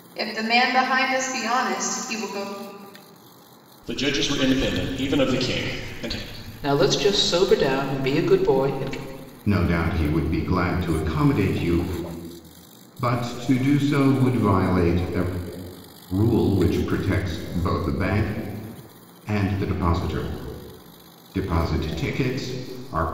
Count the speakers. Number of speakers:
four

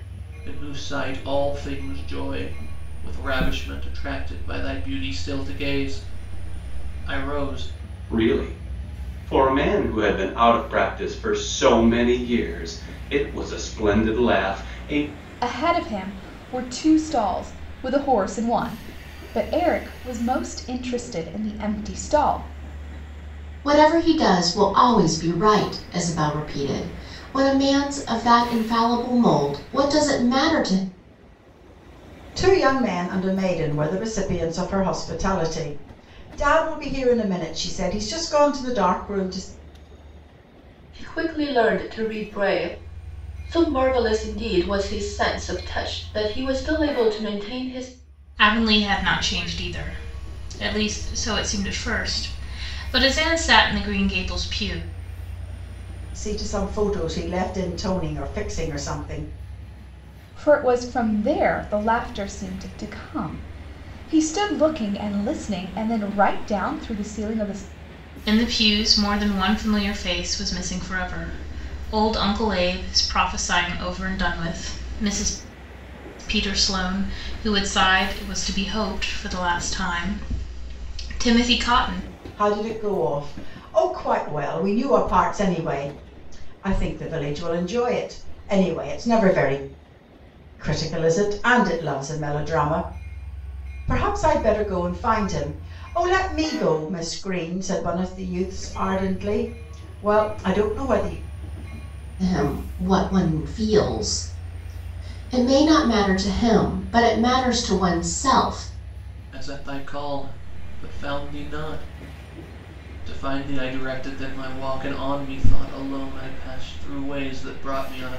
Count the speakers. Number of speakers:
seven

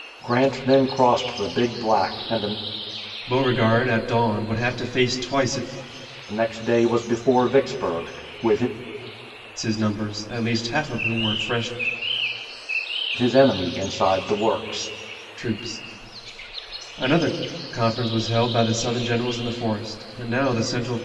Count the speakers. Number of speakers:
two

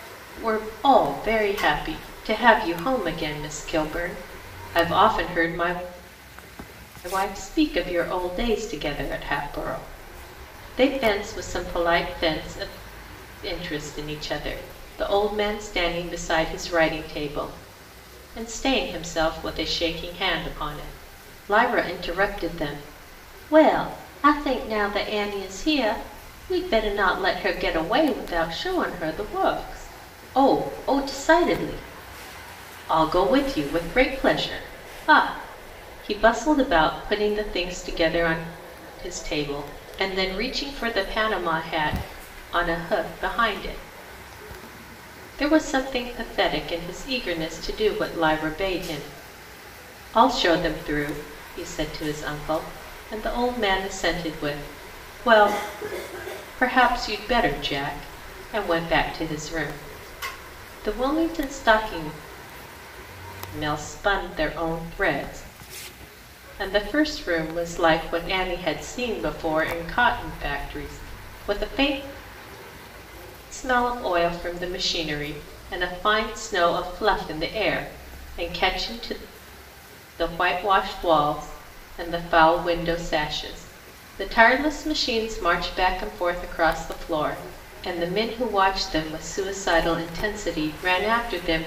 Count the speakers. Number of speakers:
one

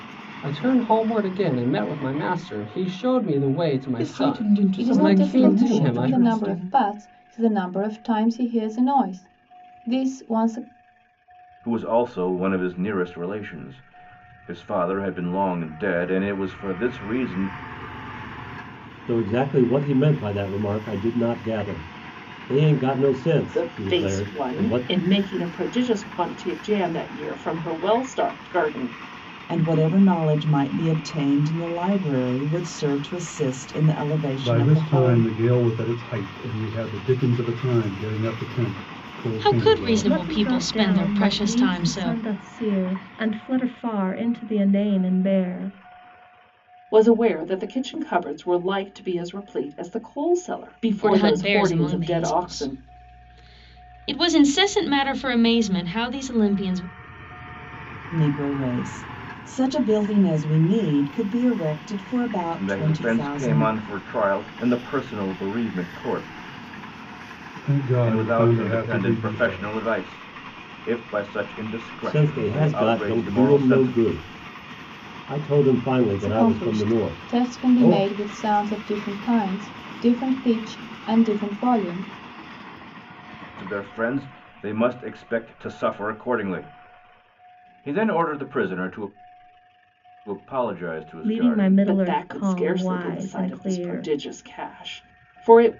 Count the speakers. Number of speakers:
ten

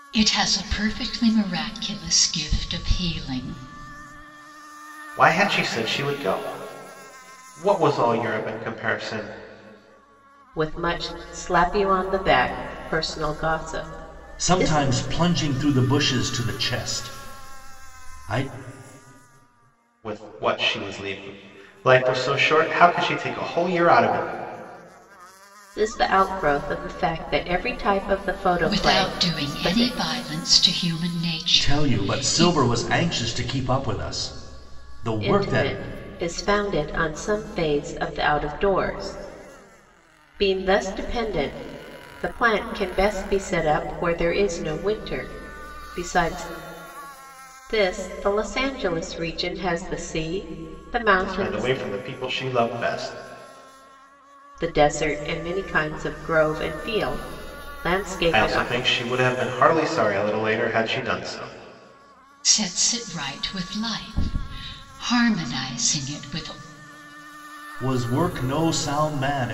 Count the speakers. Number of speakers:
four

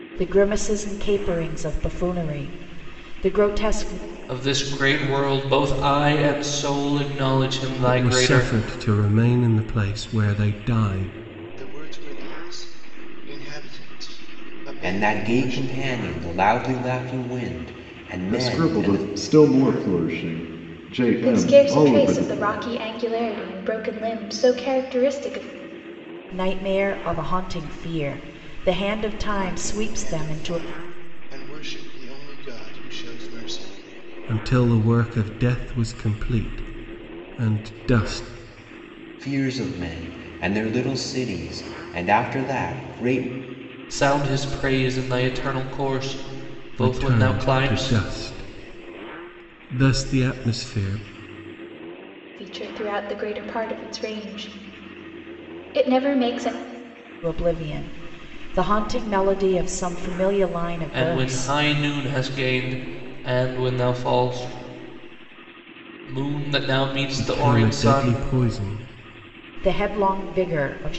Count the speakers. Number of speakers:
seven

